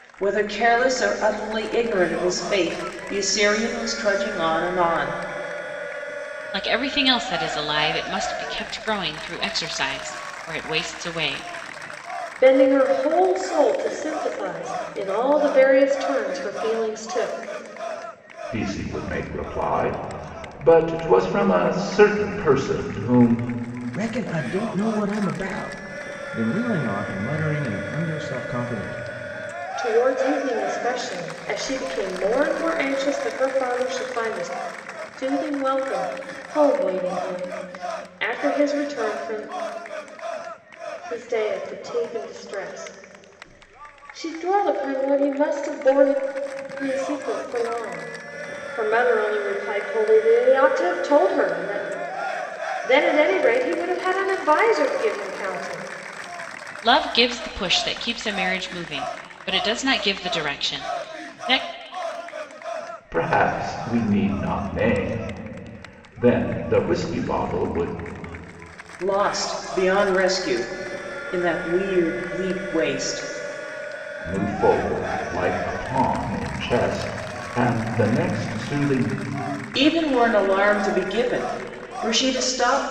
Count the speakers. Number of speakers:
5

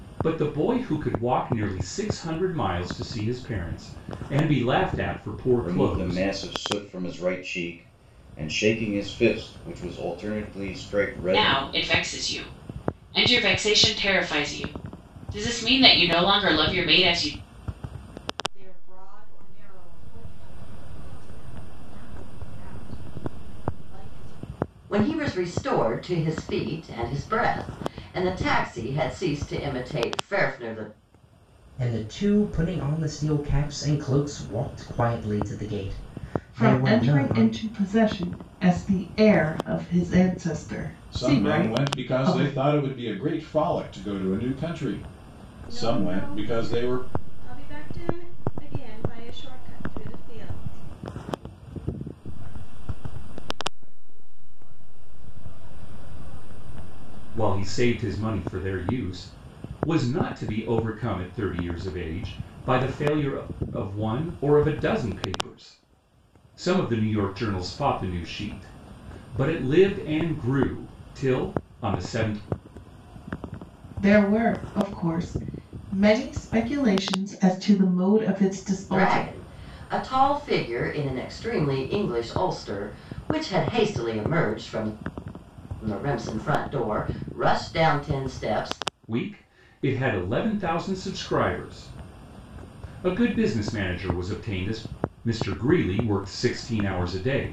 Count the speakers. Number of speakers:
10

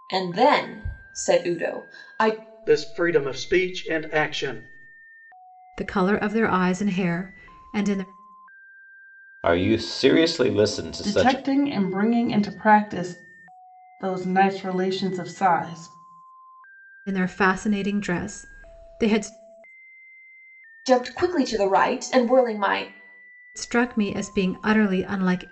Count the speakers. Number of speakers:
5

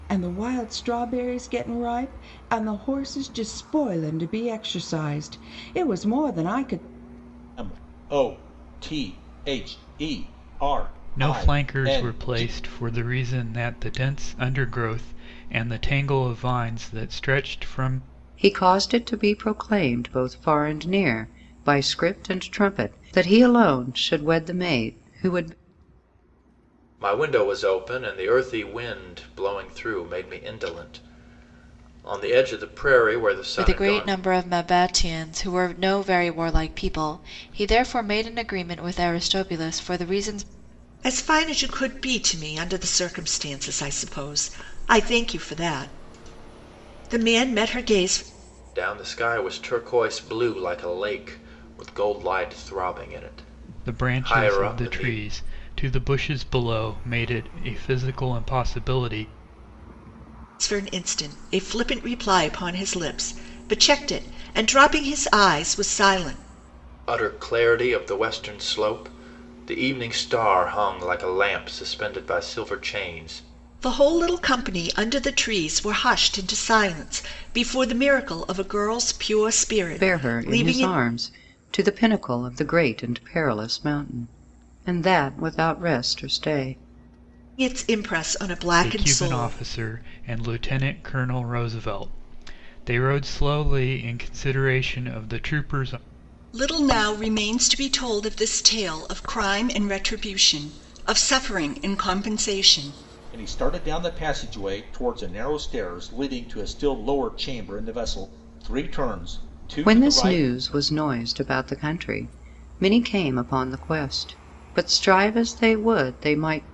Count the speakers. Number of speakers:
7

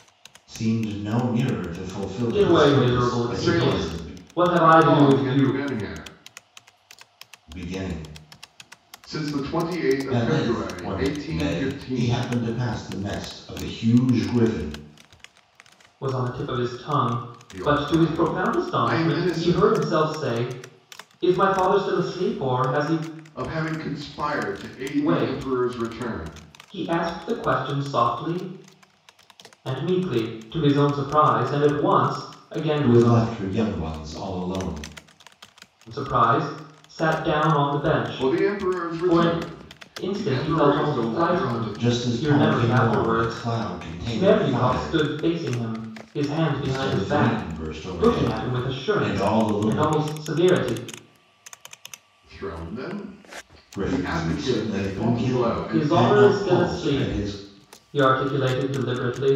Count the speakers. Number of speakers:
3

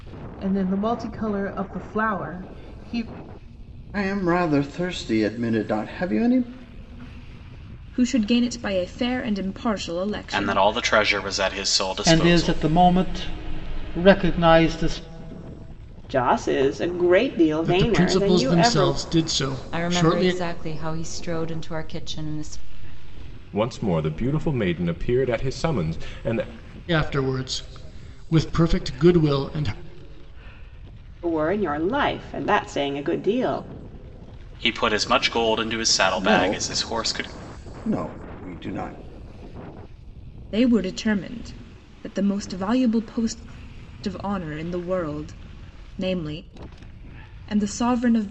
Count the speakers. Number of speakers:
9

